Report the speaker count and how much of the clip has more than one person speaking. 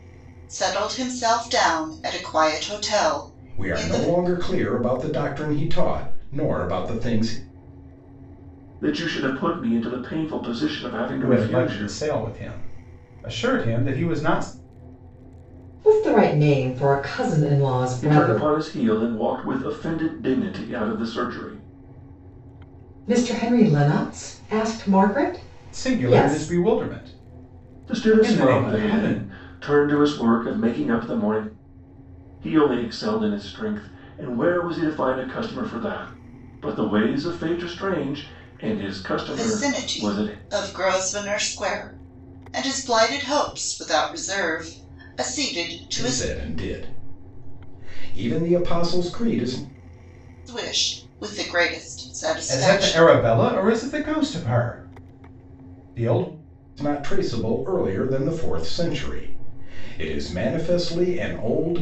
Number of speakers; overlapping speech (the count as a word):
five, about 10%